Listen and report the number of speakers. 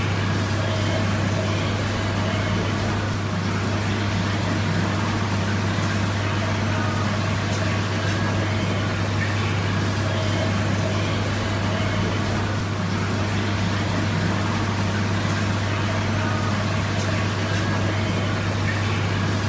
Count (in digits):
0